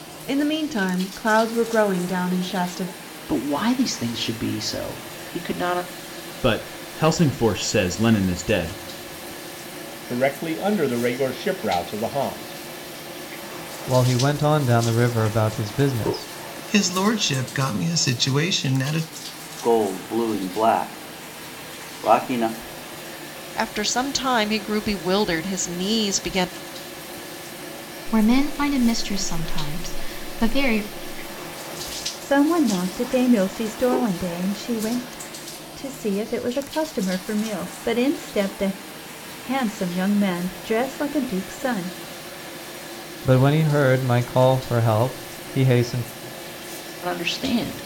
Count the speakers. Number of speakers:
10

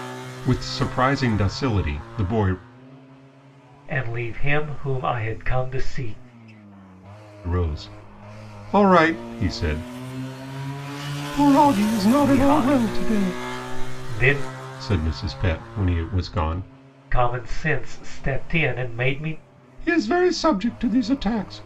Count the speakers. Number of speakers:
2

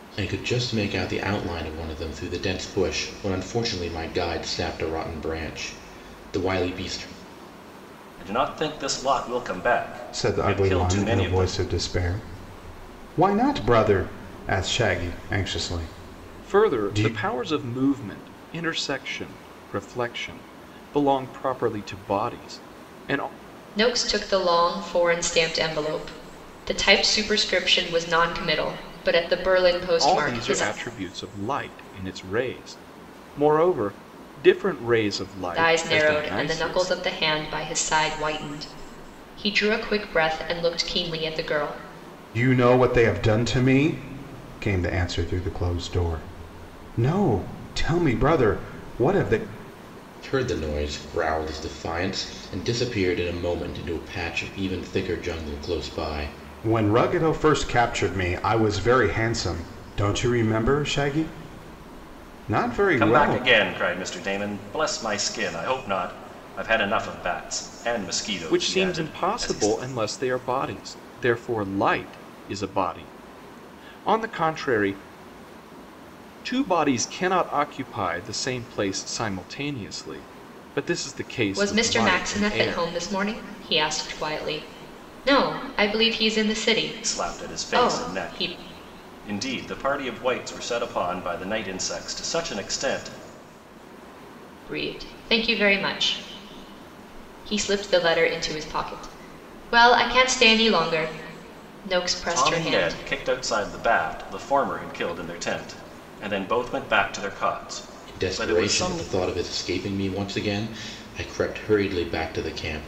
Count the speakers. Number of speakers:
5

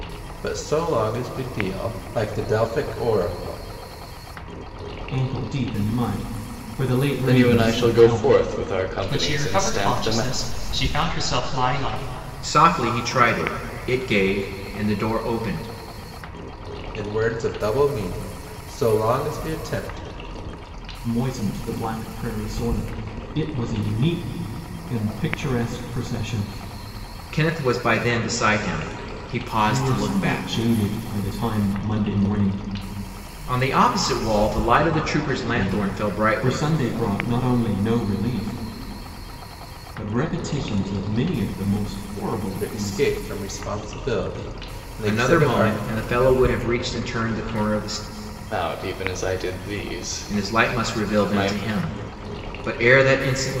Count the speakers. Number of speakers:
5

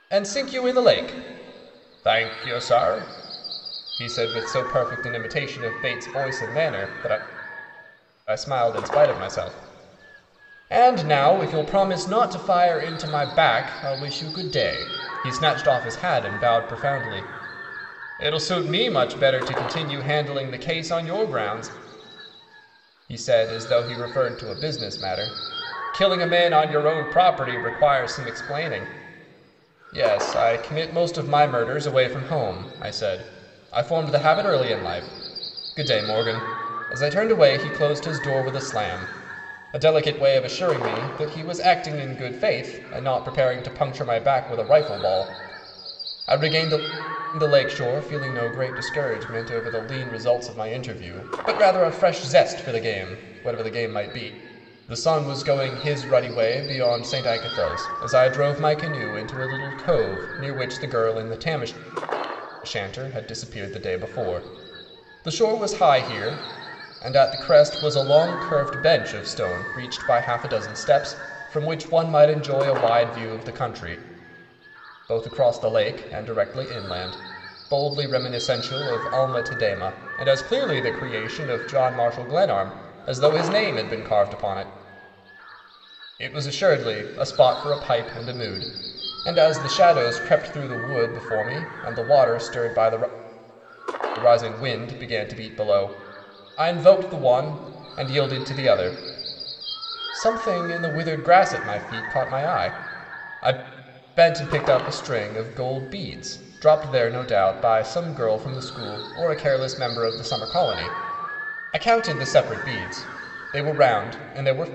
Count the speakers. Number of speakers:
1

